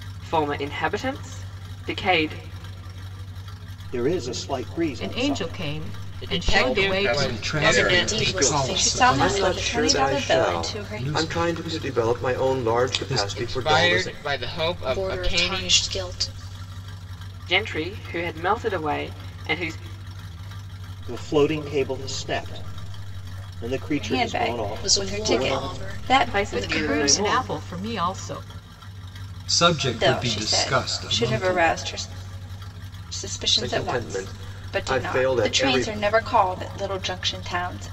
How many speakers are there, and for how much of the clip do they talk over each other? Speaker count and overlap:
9, about 45%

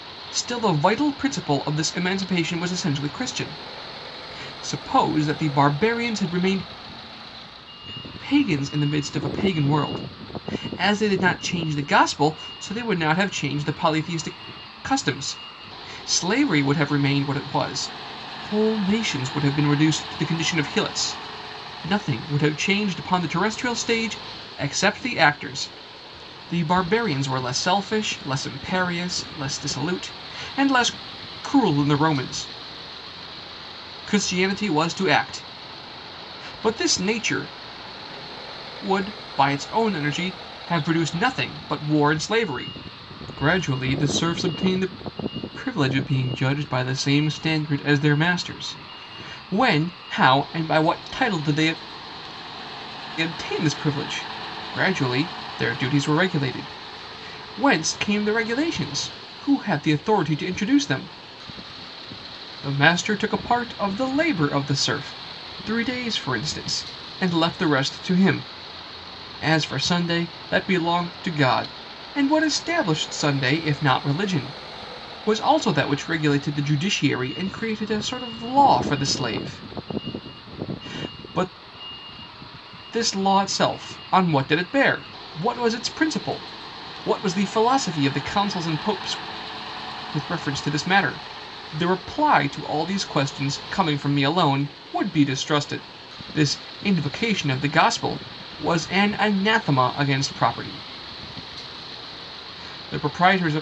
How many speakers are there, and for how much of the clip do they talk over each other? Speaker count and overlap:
1, no overlap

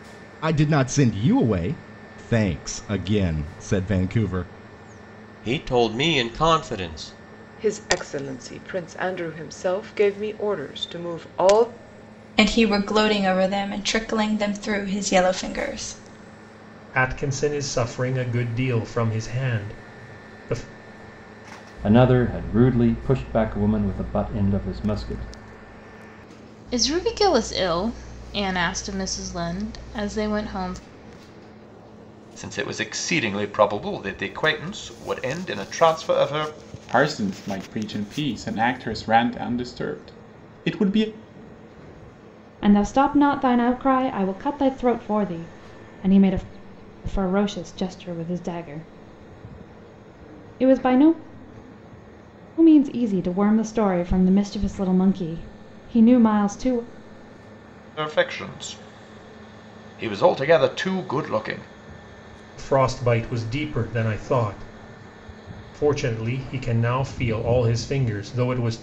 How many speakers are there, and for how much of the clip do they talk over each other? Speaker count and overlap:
10, no overlap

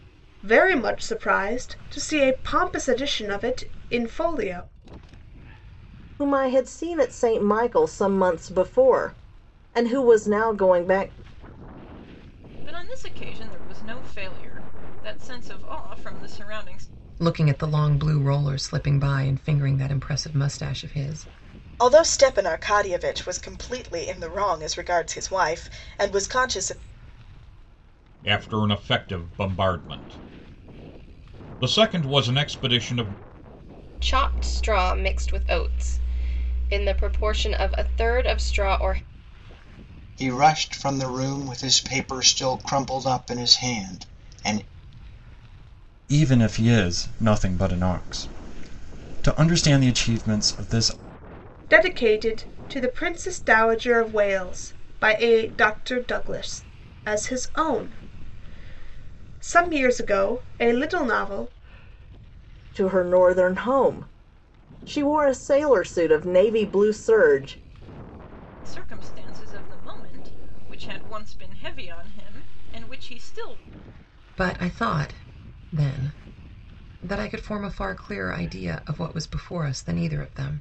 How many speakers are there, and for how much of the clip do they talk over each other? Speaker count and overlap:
9, no overlap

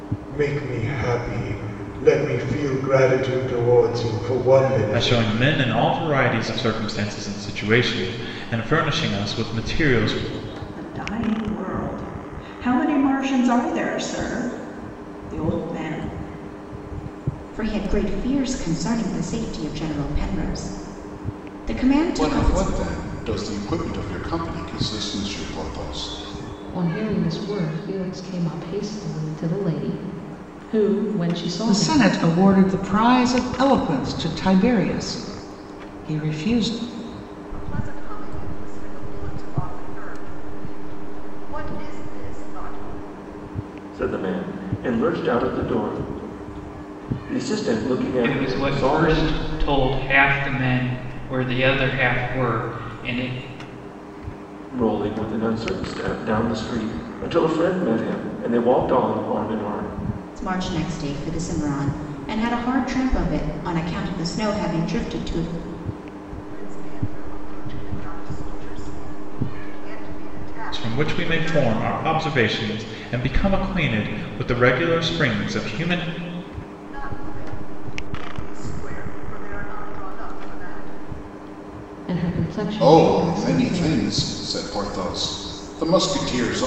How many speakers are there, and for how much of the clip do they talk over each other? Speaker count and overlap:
10, about 6%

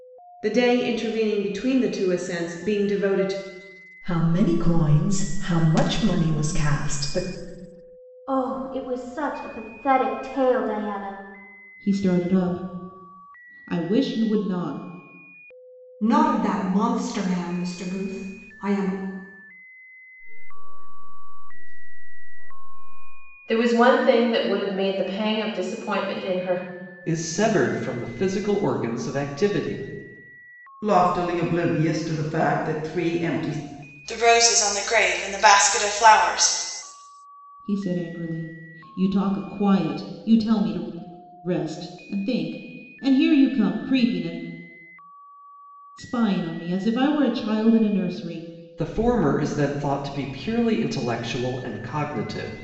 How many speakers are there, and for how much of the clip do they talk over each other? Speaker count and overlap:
10, no overlap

